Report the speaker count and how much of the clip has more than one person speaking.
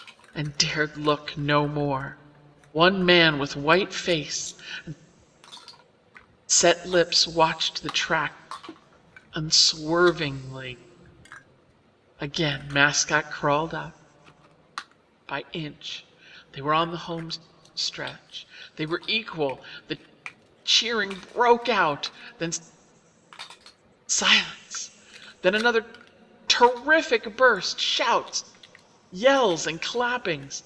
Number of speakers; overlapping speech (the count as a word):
one, no overlap